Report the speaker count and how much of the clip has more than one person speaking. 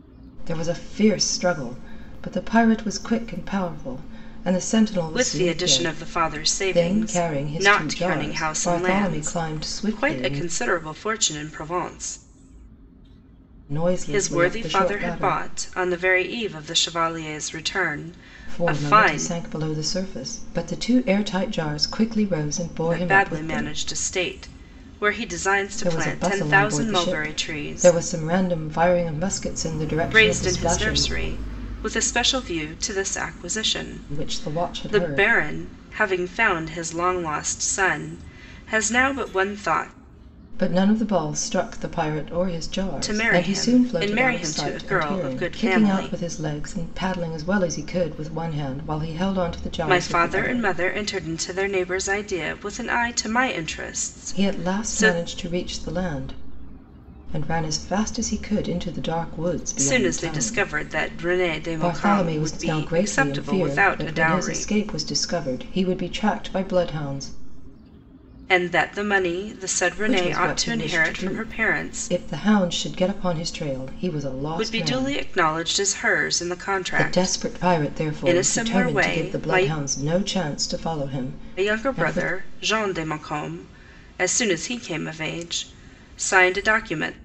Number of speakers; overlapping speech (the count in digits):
2, about 33%